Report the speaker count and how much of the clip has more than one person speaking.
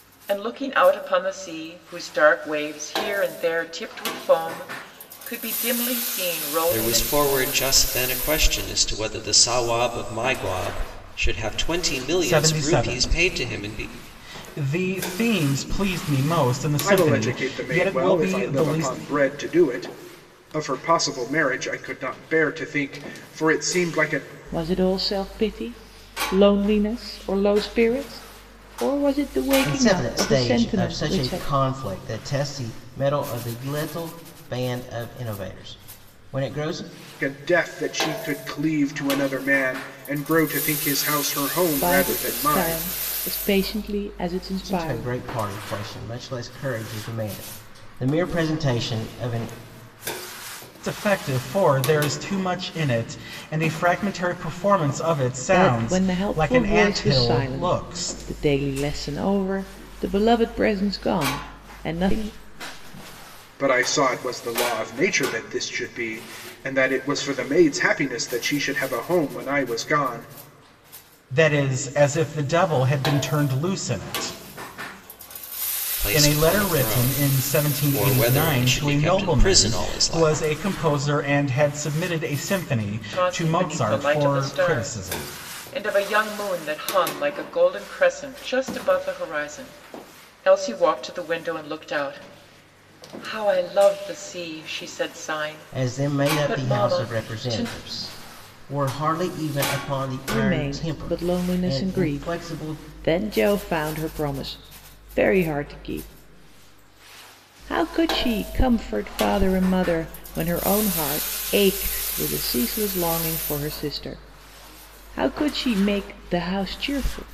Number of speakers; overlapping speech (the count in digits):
6, about 19%